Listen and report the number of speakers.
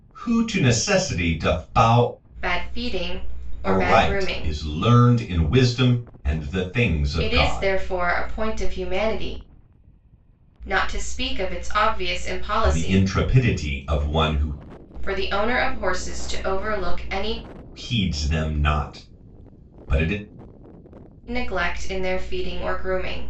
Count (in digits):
2